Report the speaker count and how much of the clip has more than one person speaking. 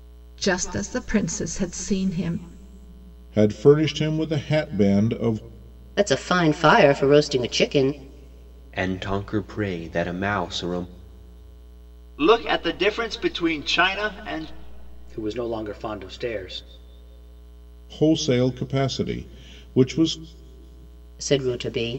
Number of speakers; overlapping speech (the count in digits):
6, no overlap